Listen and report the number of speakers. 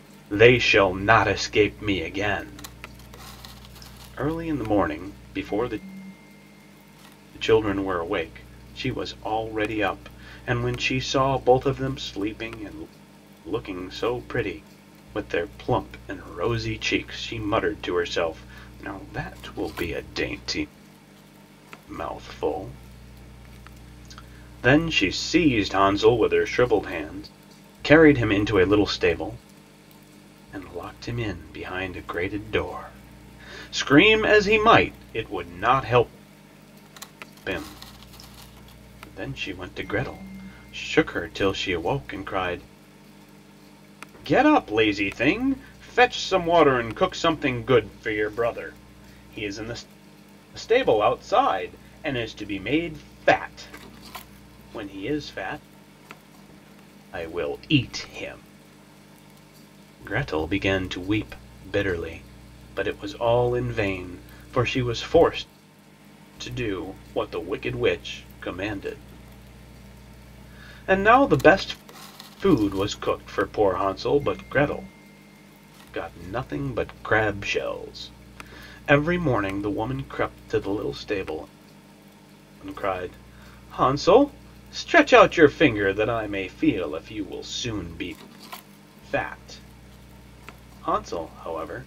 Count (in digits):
1